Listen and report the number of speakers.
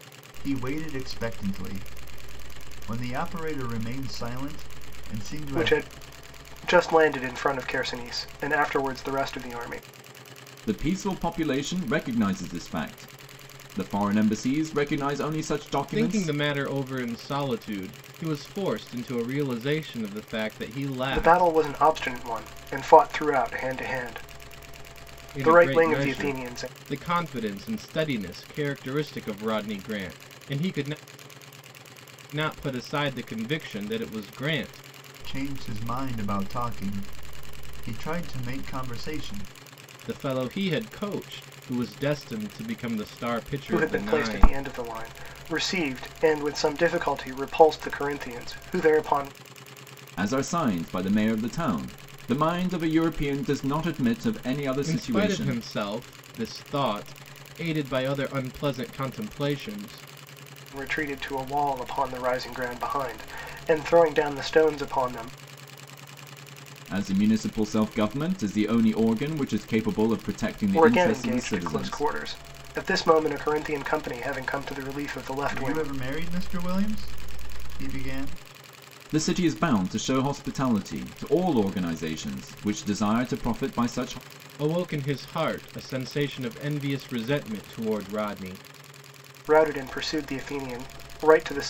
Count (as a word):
four